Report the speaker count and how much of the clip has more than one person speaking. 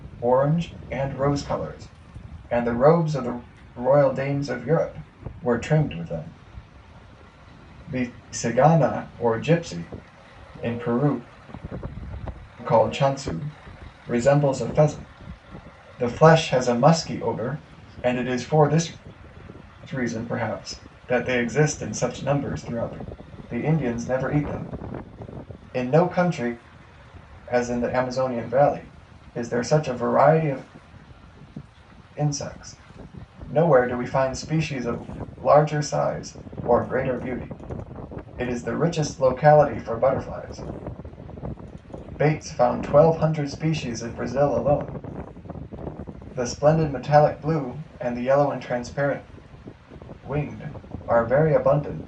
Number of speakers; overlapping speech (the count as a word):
one, no overlap